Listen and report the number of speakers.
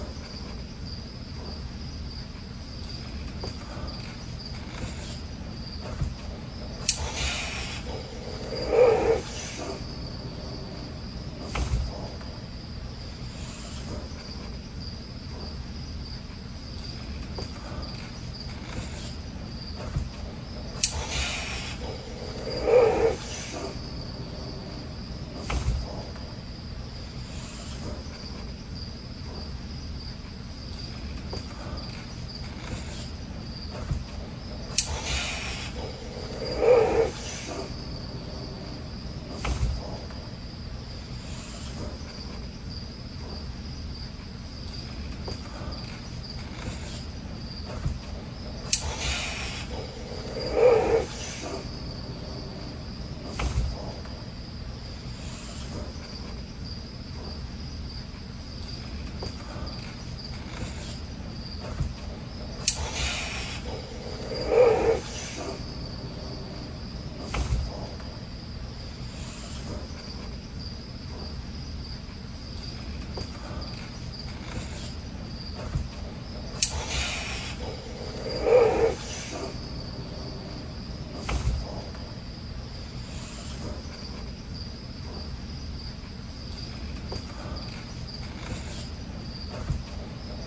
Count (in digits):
0